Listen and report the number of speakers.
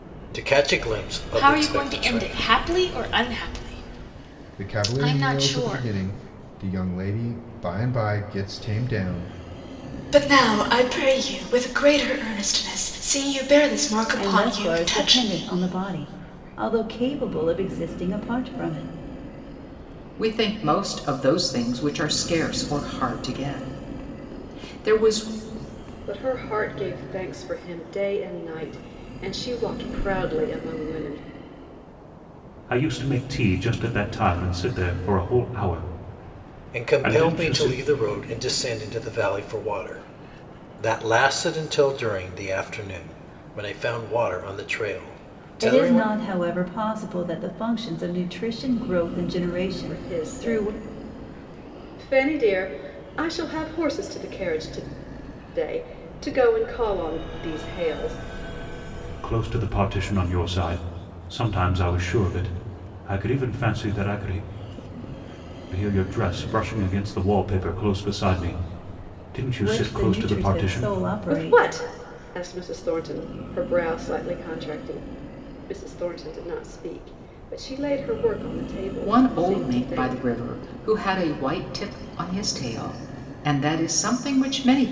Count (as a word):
eight